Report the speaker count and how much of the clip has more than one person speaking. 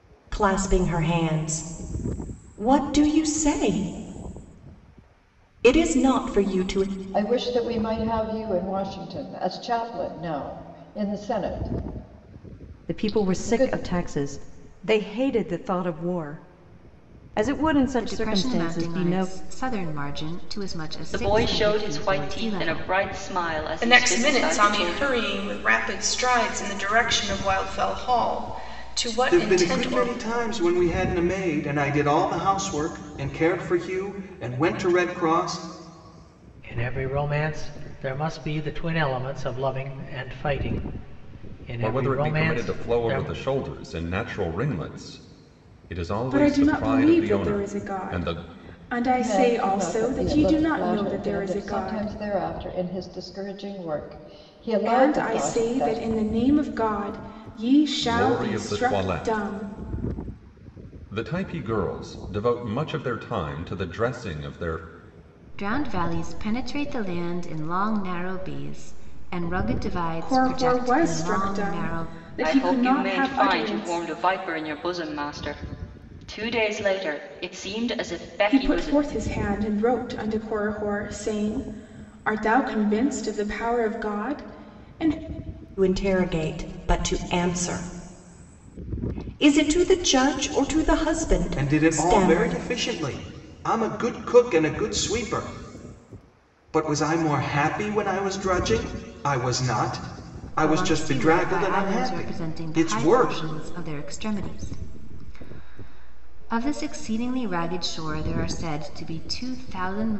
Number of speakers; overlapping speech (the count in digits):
10, about 22%